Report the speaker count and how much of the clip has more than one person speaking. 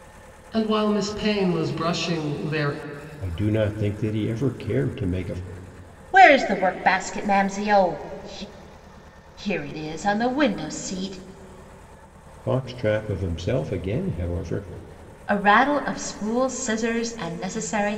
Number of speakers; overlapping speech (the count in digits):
3, no overlap